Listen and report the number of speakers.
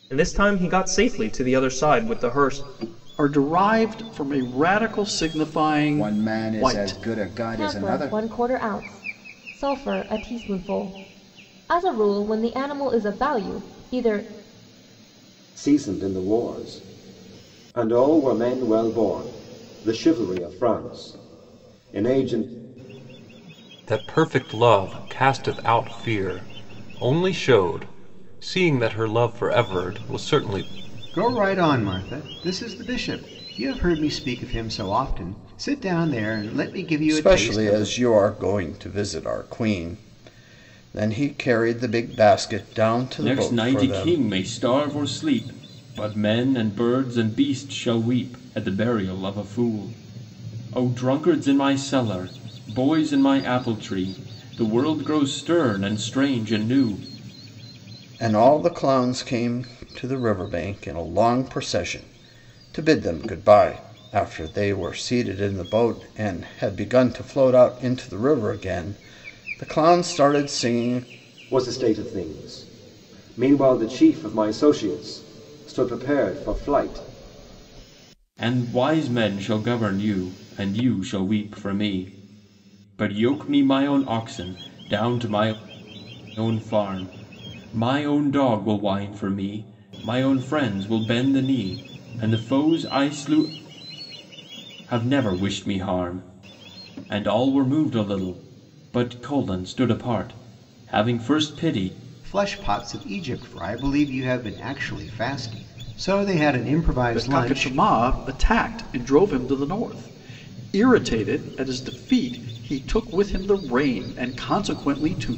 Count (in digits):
9